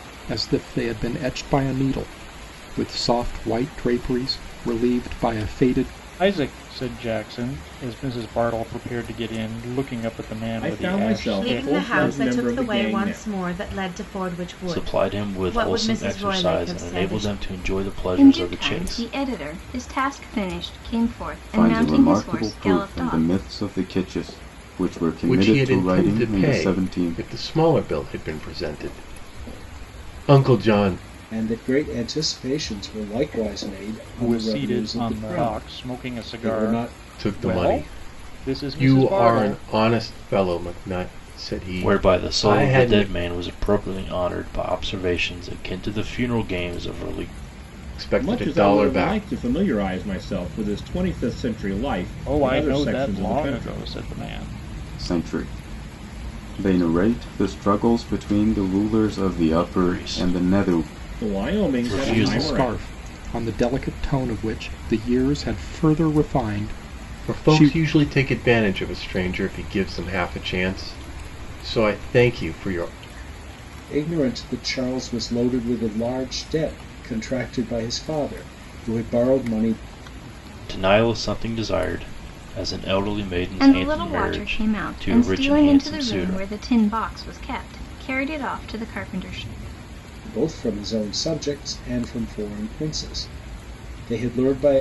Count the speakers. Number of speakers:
9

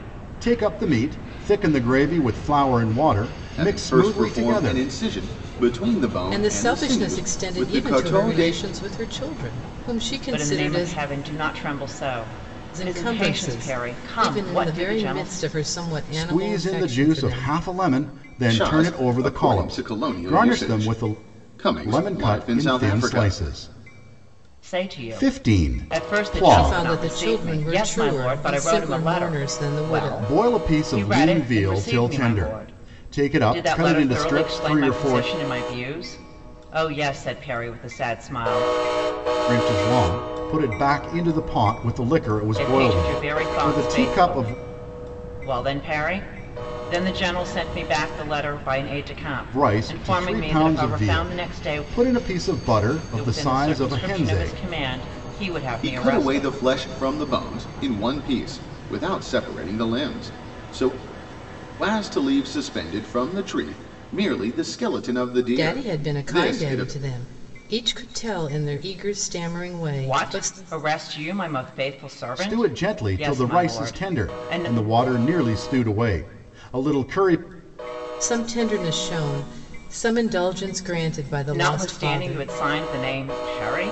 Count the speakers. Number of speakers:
4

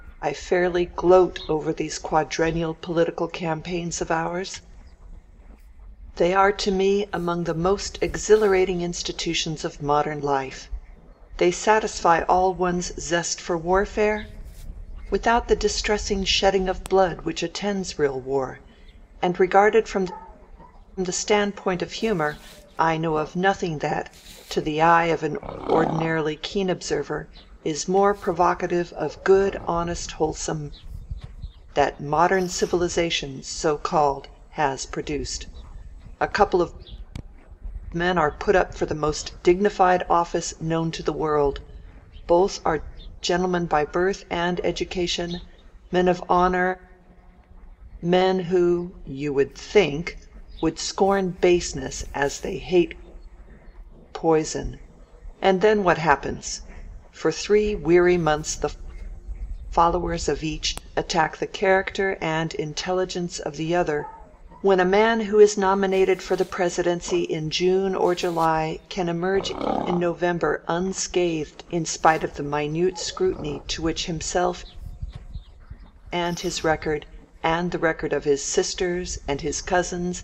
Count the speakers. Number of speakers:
1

